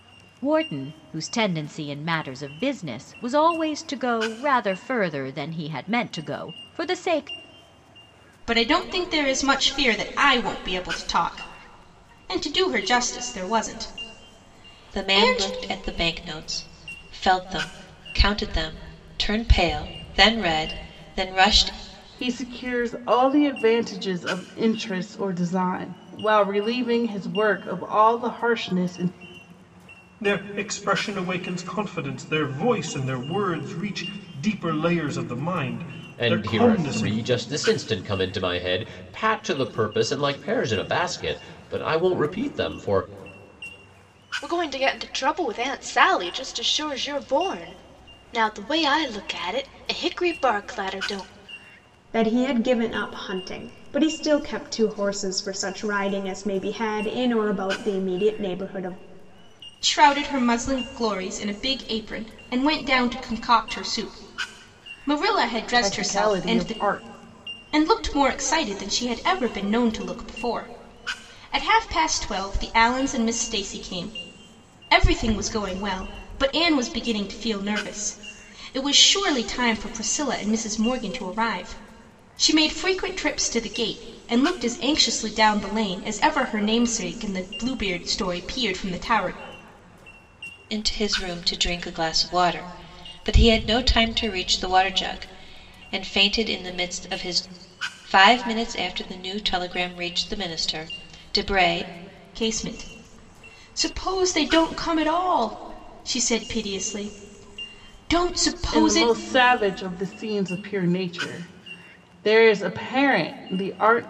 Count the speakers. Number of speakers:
8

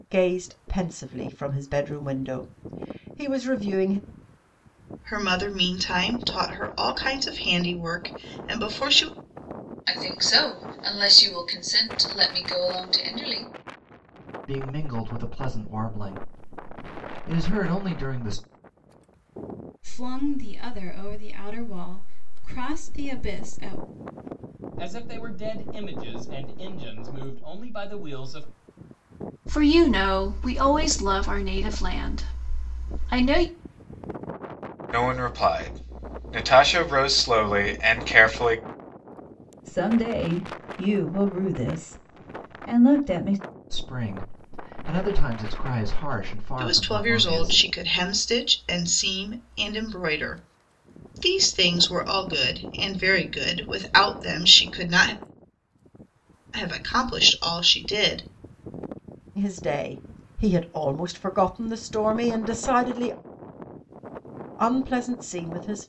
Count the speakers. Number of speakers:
9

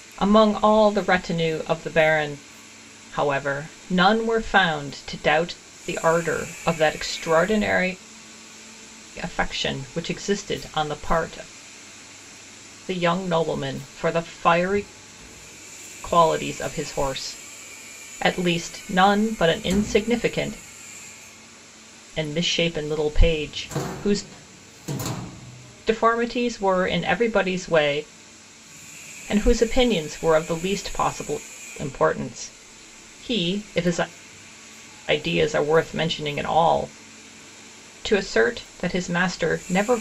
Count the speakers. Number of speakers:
1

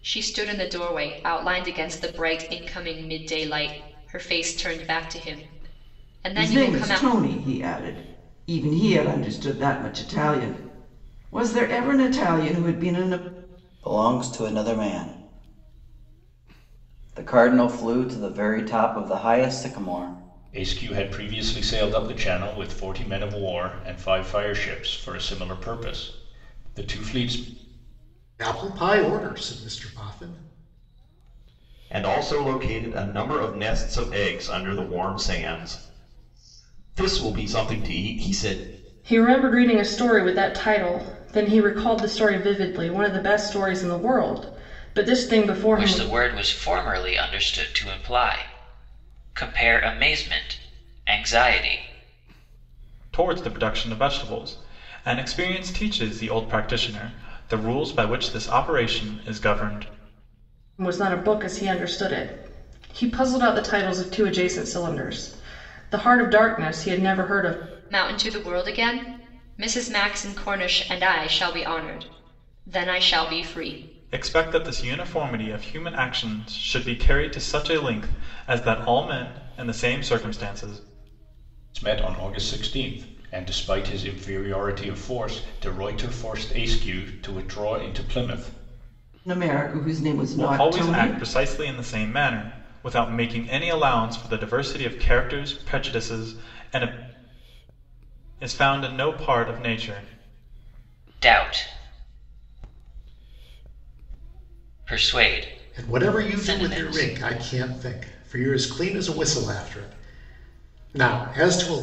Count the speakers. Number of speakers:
9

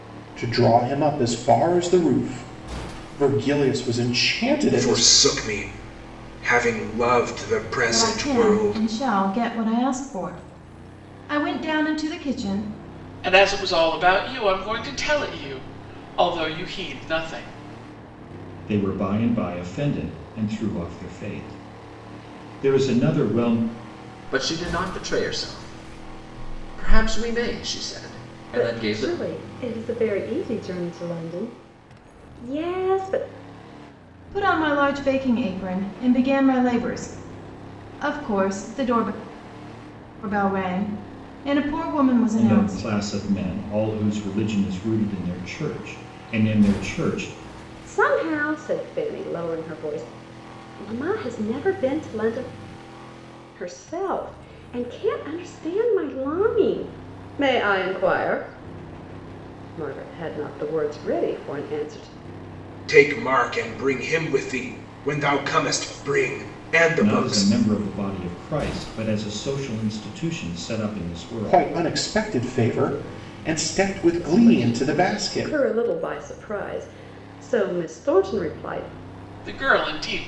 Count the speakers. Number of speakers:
7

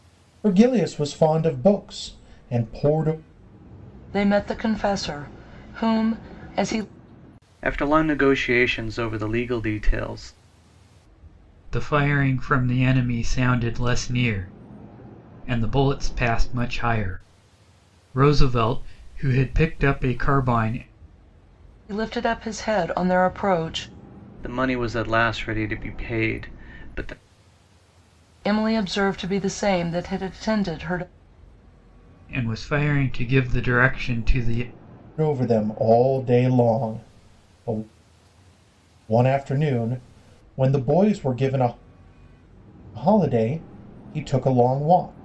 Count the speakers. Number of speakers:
4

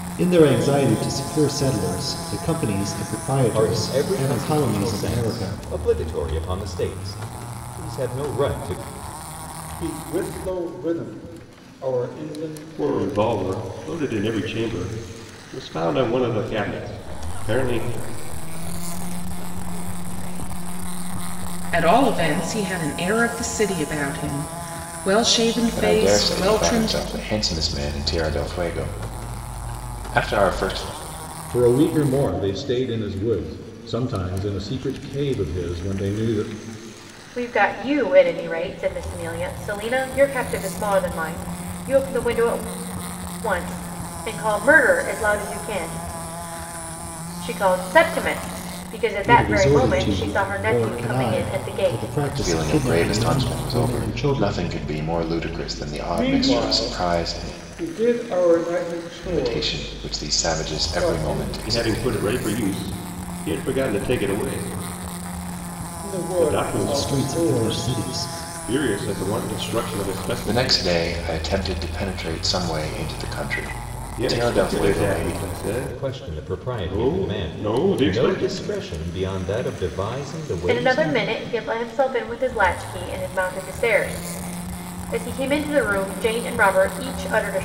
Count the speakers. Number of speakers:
9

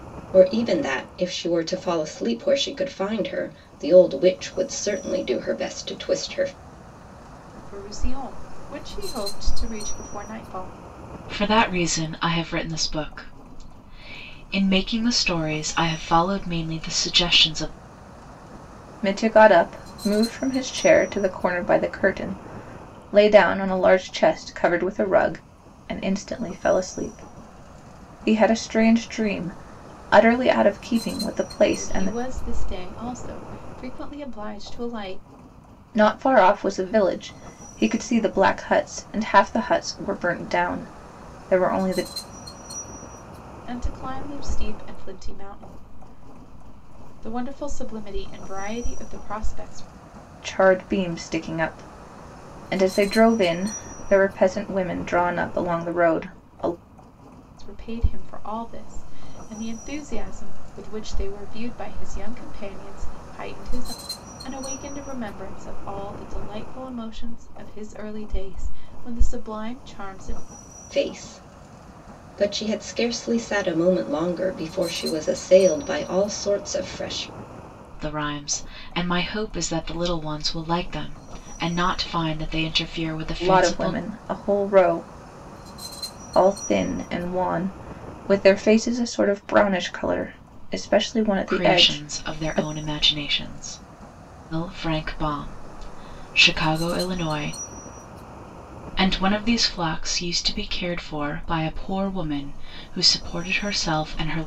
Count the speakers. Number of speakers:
4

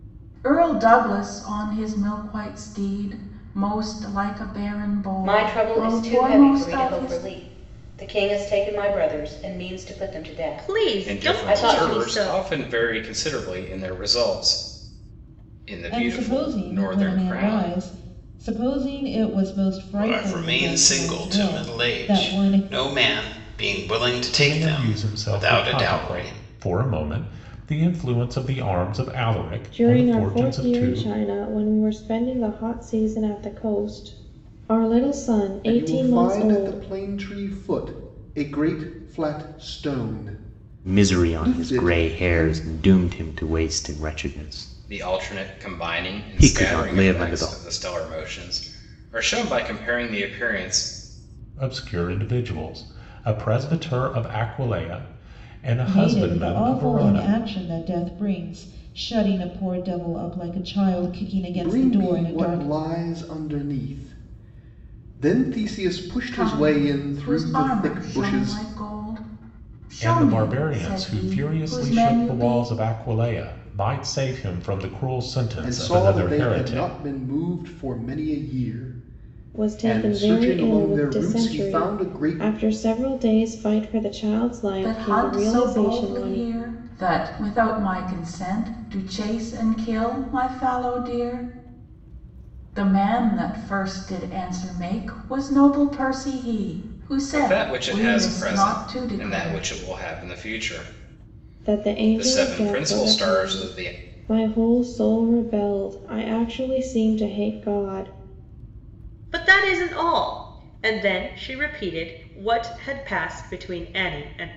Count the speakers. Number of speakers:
10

